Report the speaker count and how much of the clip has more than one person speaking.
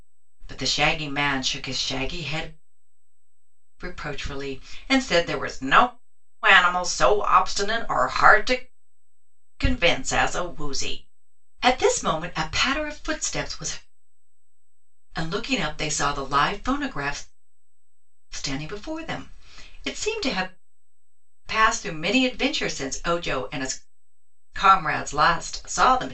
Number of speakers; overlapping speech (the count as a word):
one, no overlap